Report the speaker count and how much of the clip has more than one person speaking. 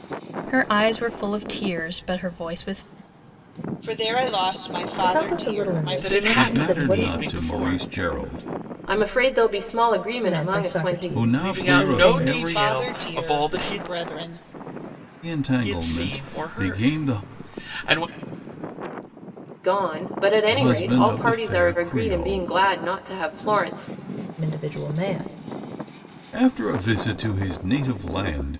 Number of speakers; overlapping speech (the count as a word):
six, about 35%